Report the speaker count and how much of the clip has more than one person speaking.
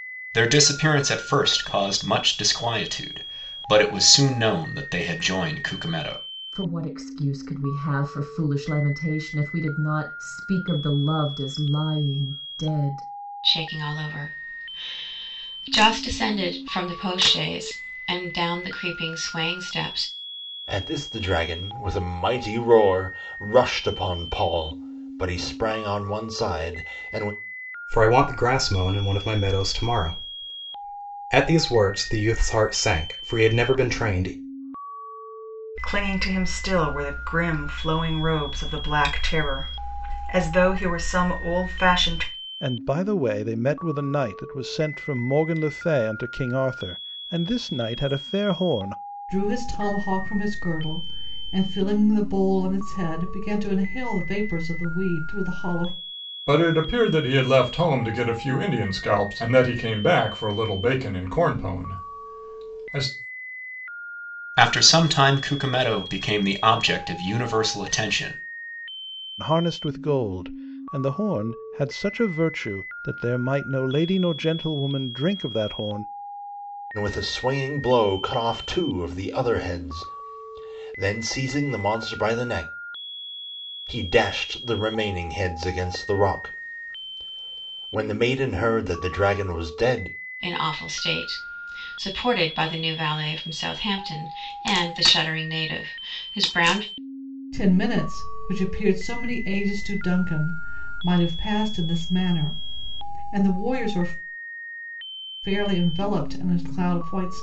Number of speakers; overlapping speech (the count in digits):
9, no overlap